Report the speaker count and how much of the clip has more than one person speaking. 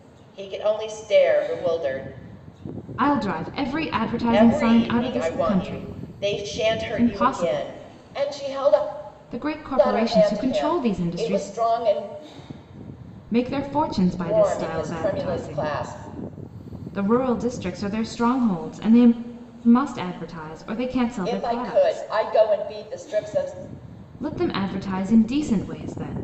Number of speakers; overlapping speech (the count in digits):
2, about 29%